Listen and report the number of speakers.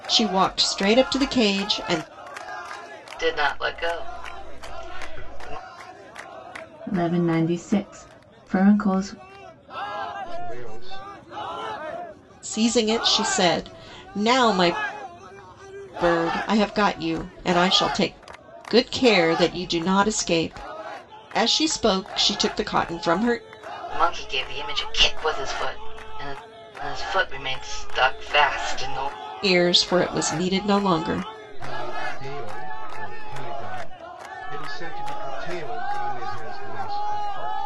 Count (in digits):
4